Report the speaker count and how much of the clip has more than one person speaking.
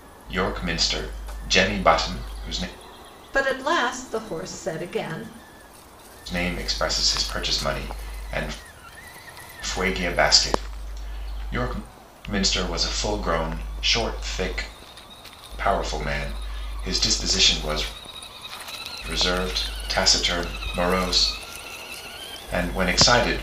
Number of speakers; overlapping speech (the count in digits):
2, no overlap